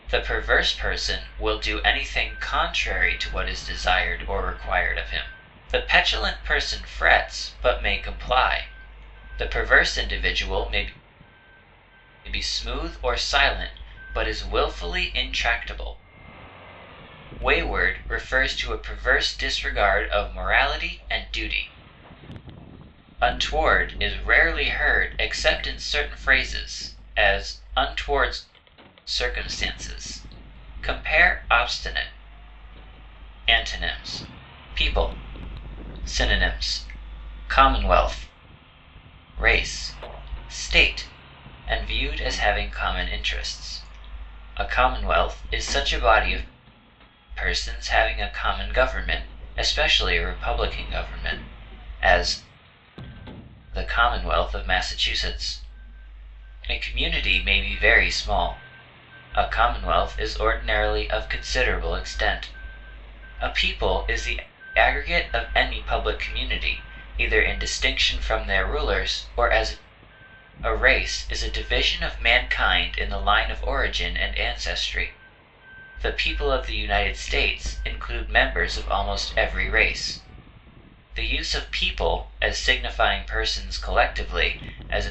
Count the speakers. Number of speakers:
1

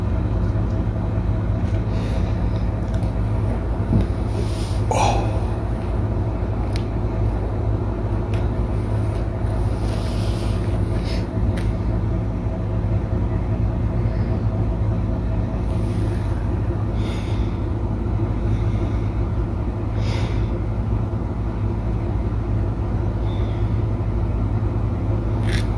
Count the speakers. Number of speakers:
0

